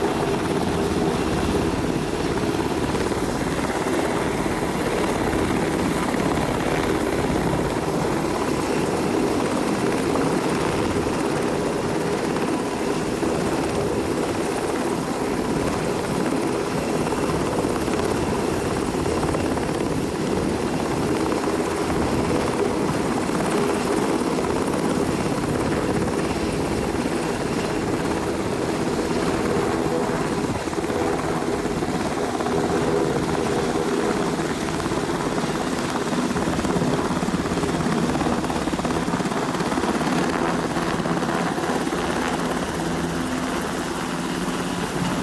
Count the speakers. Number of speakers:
zero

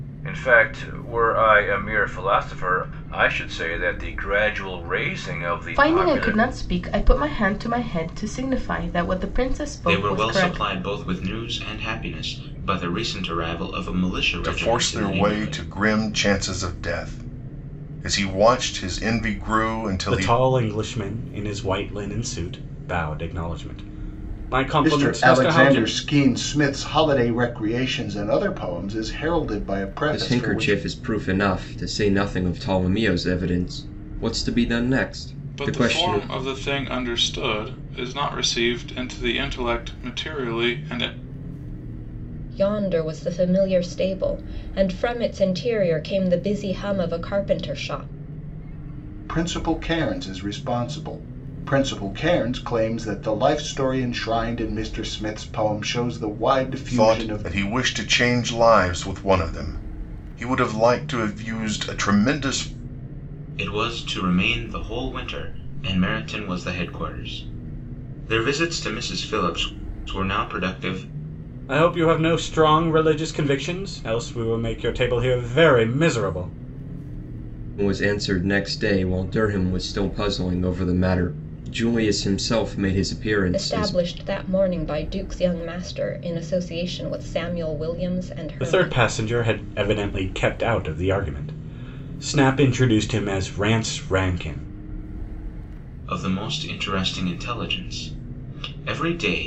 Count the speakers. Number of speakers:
nine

